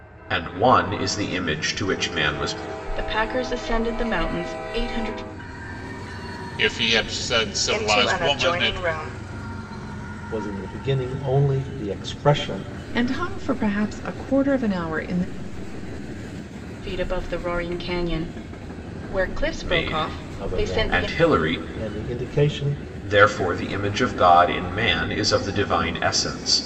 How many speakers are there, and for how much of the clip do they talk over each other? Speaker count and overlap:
6, about 12%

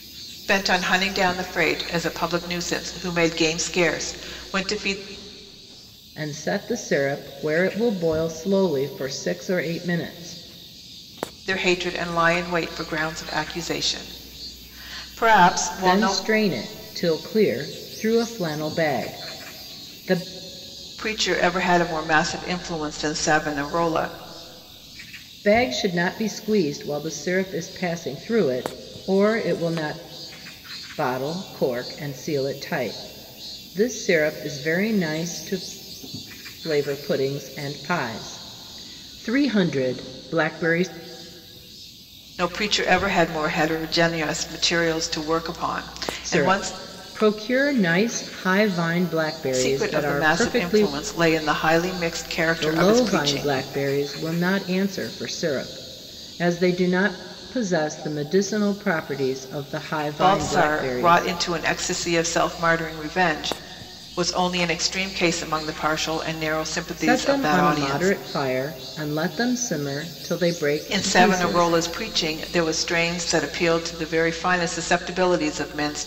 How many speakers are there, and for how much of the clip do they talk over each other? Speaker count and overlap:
2, about 9%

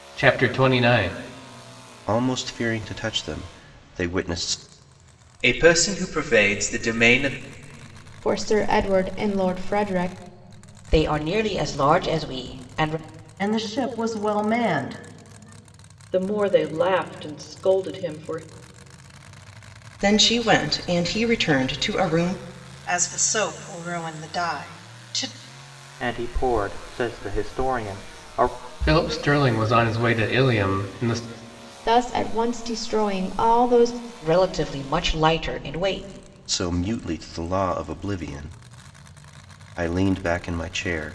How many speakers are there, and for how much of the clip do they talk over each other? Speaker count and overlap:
10, no overlap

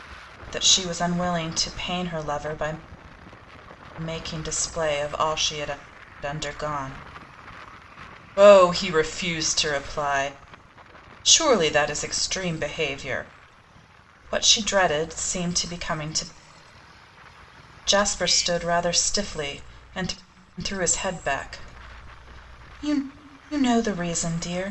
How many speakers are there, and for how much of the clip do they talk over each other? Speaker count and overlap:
1, no overlap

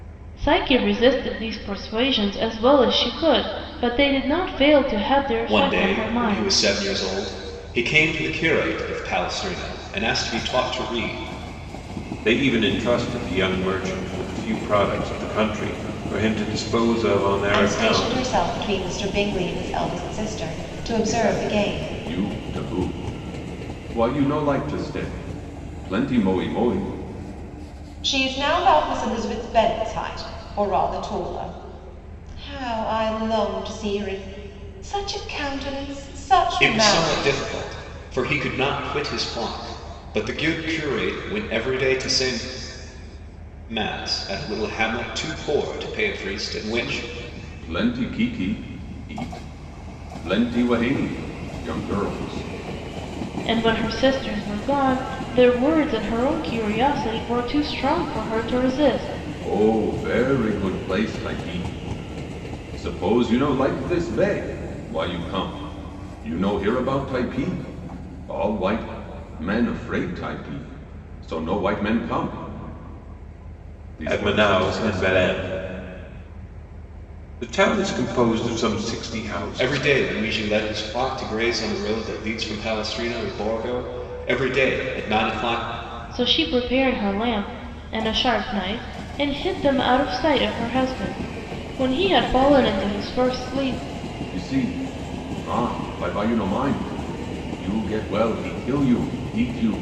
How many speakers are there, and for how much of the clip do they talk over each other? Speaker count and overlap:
5, about 6%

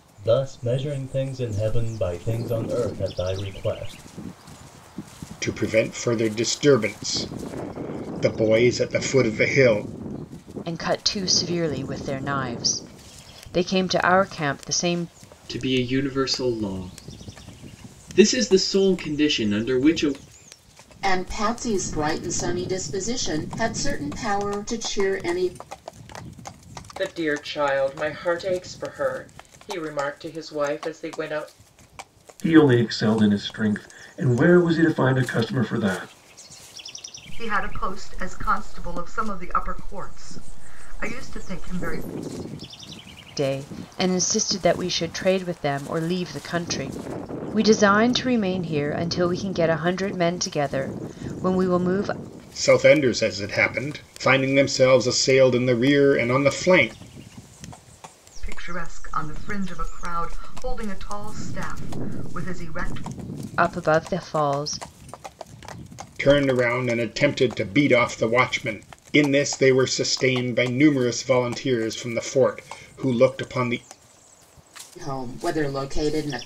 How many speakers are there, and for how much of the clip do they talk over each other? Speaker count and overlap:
8, no overlap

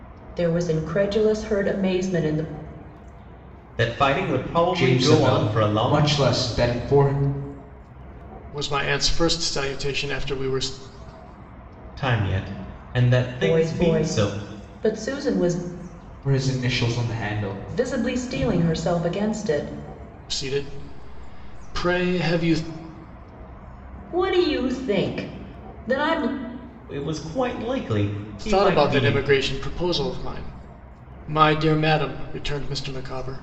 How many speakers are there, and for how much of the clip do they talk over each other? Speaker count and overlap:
4, about 12%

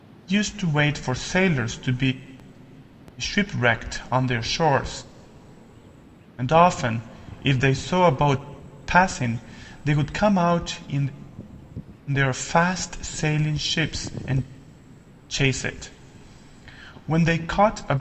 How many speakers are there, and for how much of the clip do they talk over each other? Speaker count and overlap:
1, no overlap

